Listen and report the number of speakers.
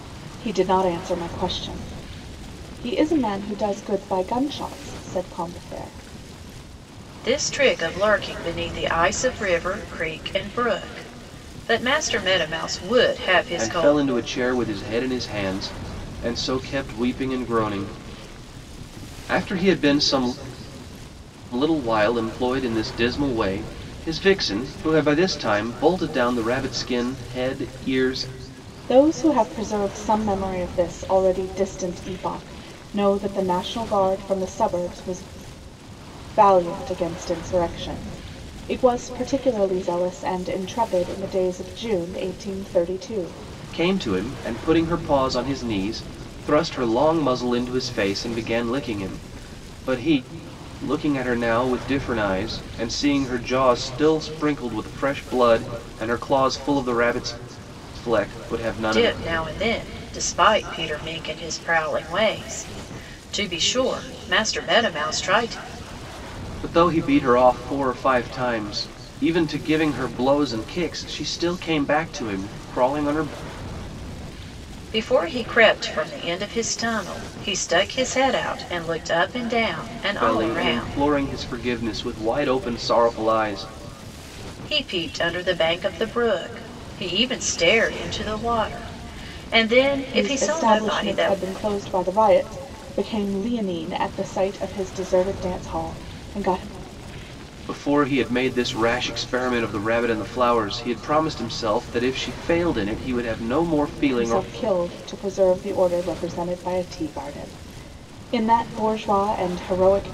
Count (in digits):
3